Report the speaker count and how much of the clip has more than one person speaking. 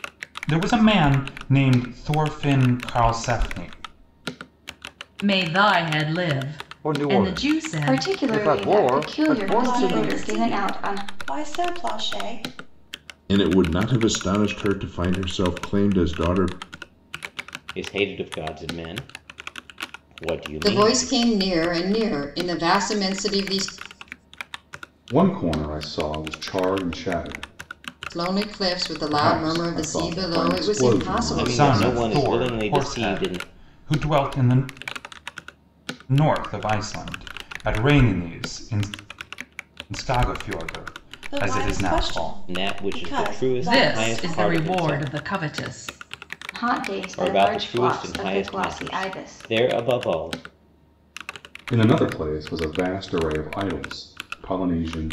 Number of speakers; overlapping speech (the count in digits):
9, about 28%